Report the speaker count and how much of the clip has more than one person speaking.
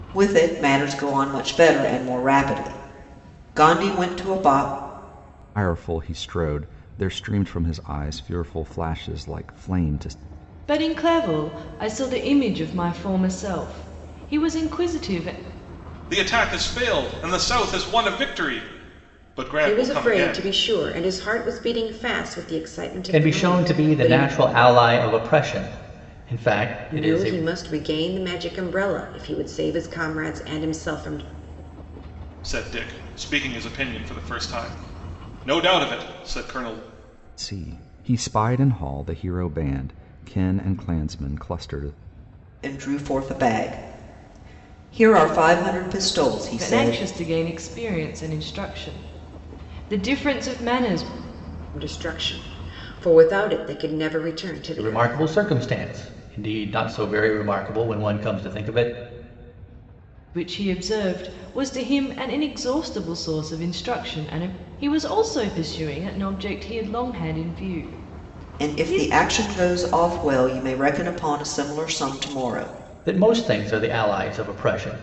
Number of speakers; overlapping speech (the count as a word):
six, about 6%